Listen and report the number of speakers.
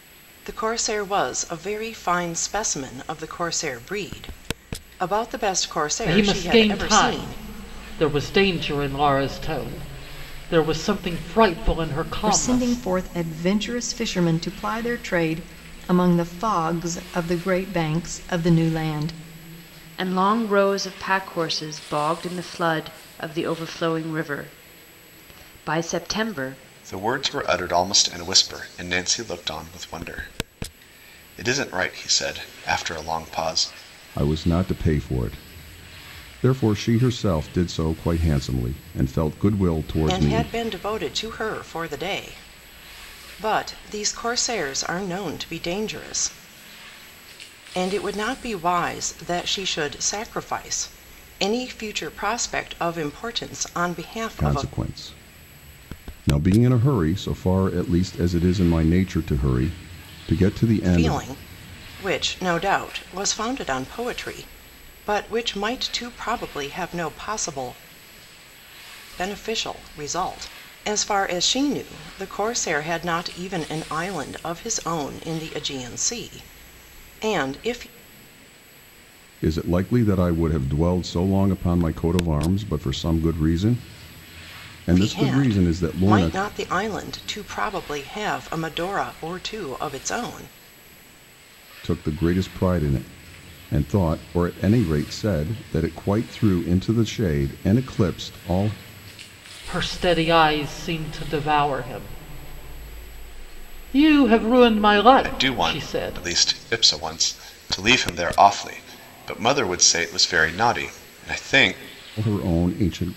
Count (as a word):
six